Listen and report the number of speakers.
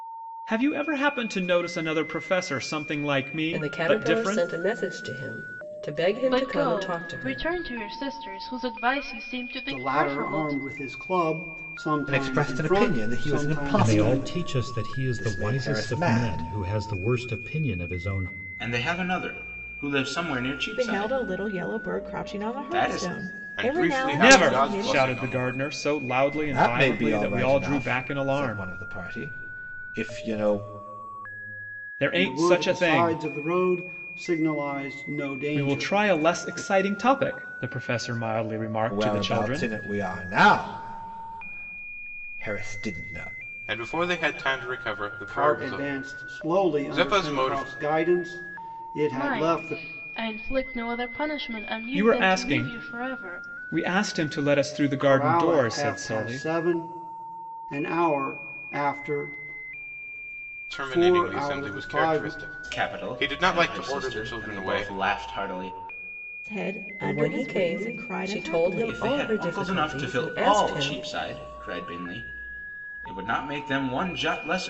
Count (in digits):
9